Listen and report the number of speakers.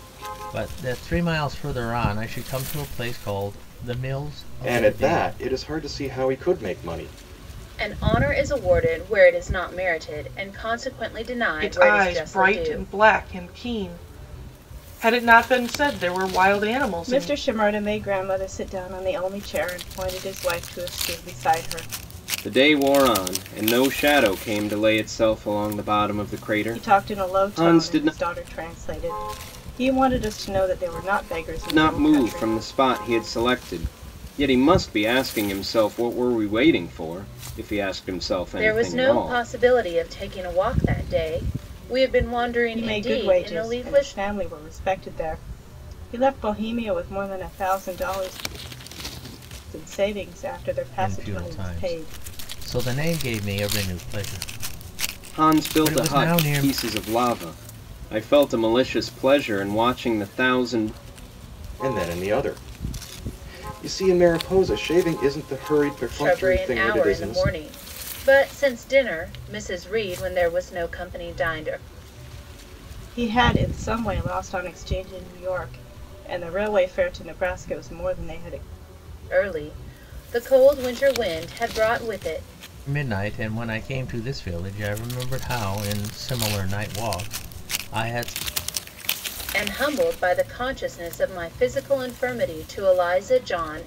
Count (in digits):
6